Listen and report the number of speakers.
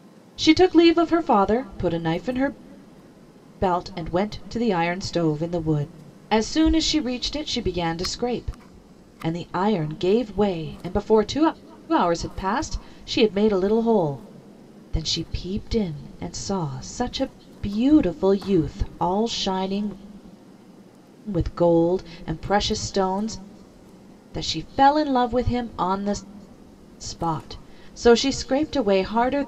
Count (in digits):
1